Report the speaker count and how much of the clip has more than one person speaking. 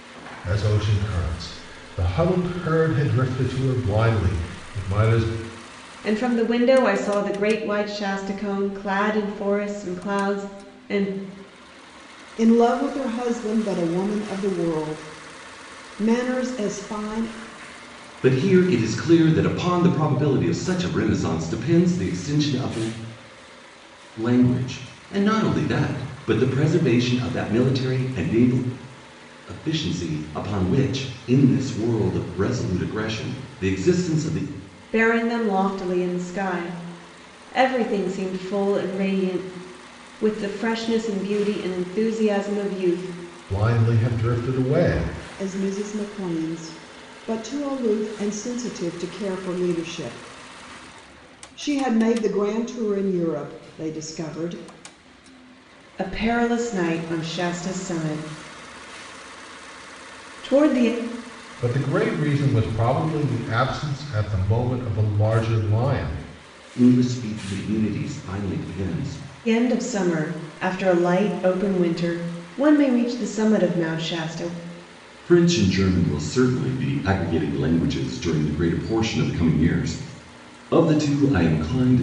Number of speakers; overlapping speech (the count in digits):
4, no overlap